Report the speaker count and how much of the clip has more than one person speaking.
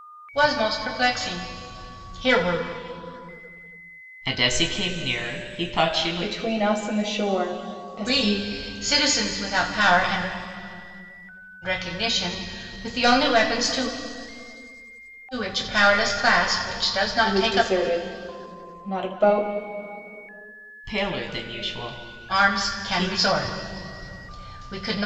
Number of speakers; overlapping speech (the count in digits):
3, about 9%